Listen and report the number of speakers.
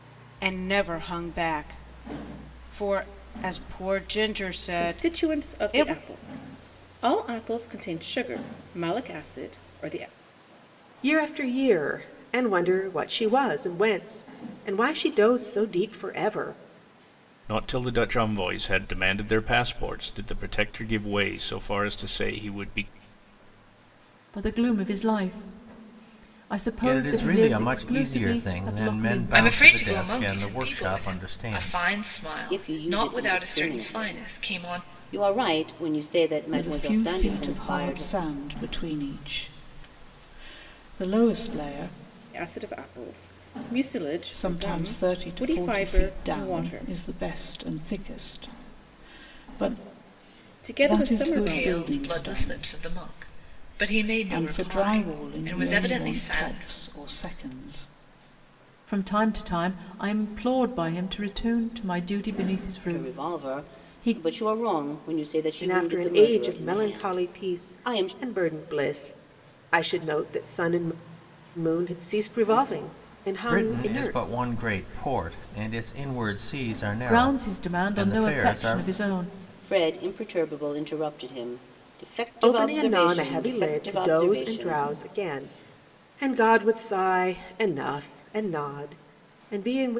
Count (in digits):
9